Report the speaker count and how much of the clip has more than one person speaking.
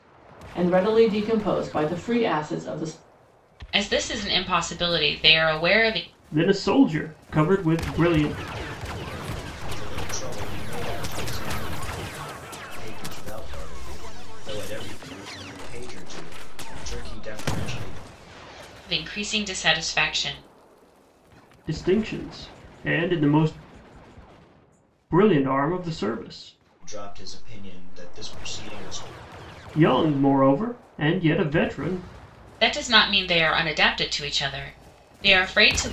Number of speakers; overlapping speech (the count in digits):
4, no overlap